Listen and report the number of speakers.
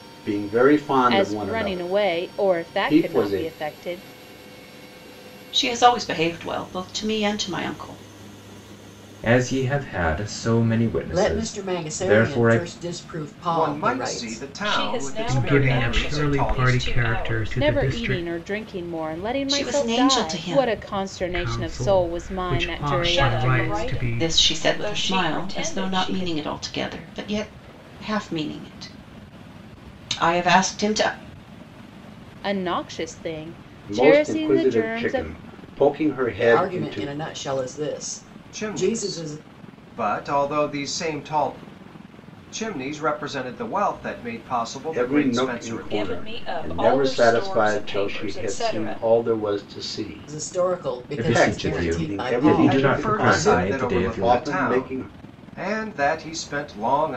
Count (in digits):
8